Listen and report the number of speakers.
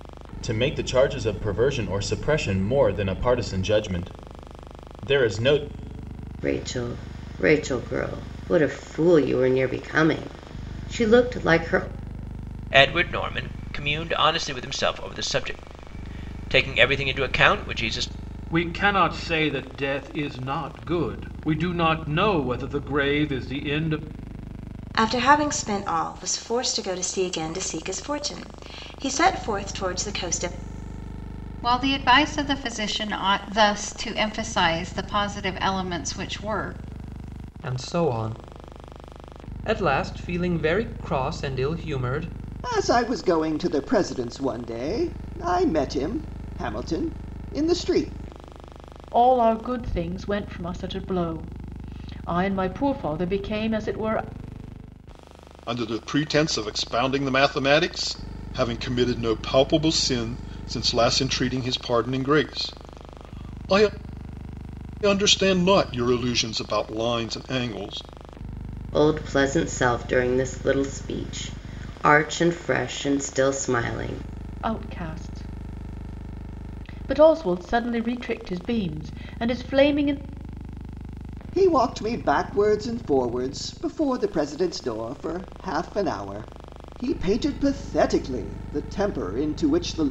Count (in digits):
10